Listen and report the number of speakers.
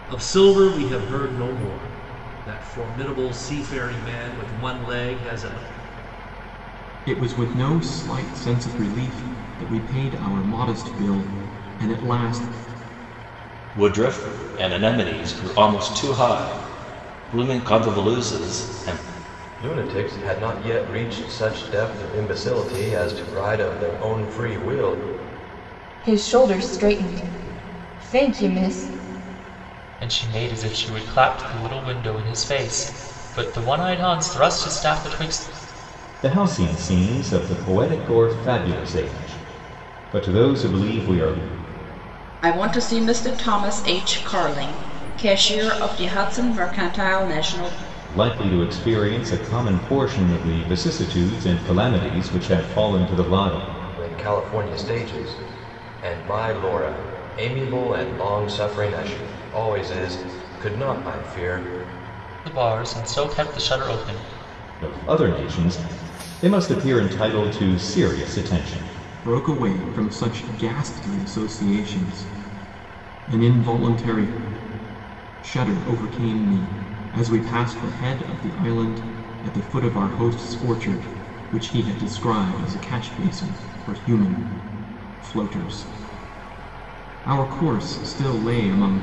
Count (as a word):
eight